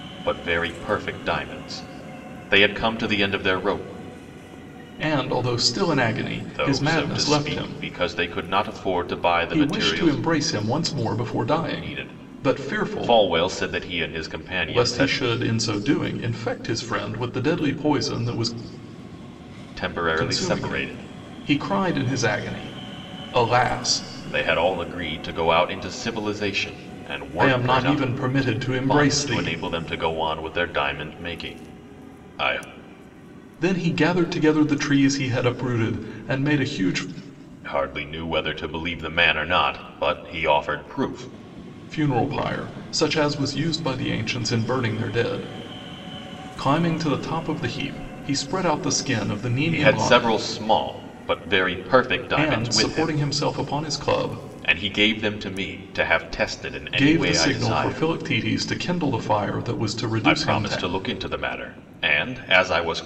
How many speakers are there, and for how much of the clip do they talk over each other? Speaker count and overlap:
two, about 16%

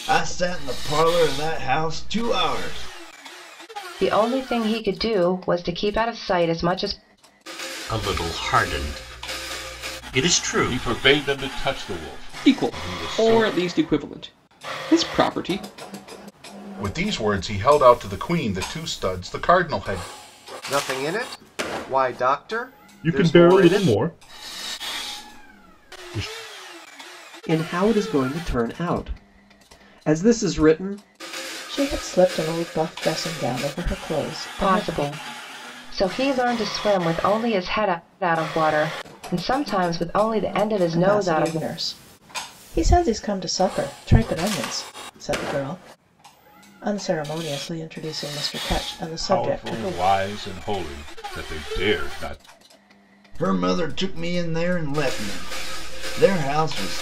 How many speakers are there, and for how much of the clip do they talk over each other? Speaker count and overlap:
ten, about 8%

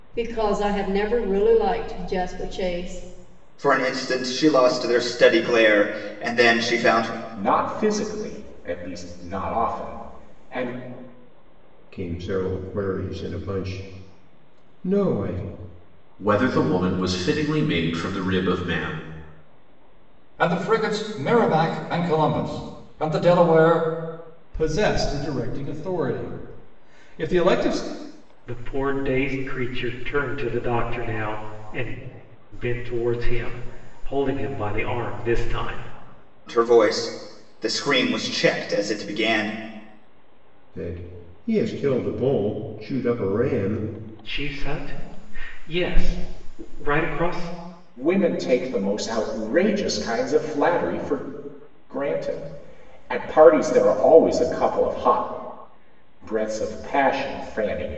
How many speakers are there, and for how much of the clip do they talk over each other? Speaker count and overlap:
eight, no overlap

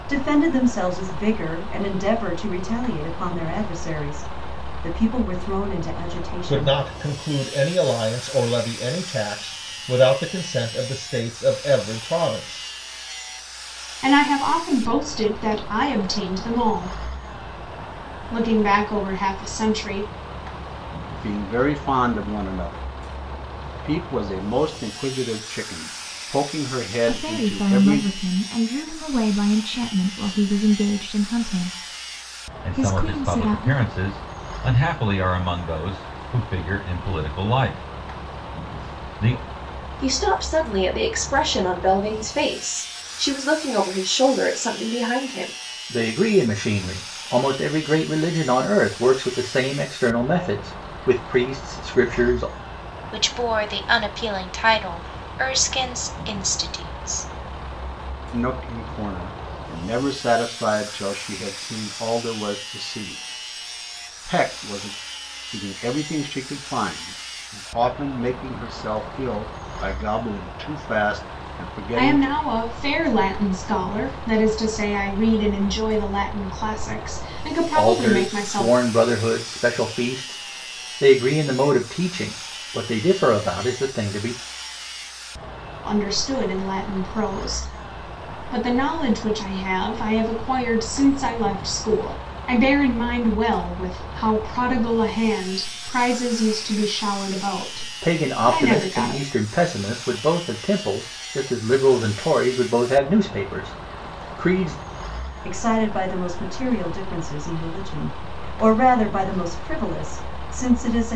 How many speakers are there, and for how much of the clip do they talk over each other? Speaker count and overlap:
nine, about 5%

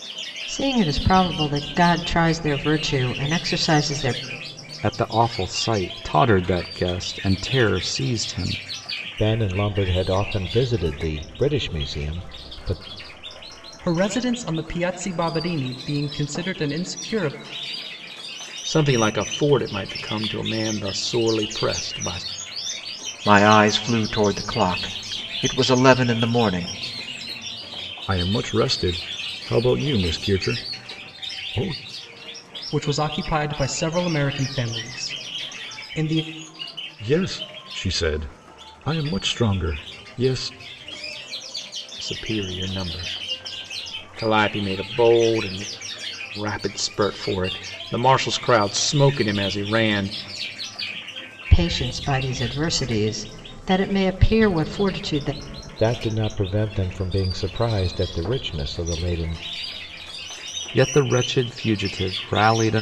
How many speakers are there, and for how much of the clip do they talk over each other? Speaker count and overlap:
seven, no overlap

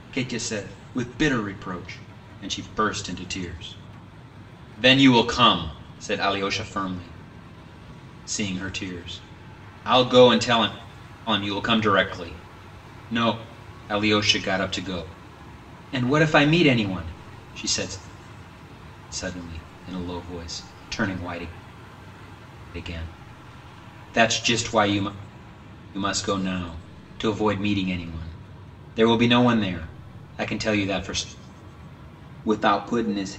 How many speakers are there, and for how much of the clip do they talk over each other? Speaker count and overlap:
one, no overlap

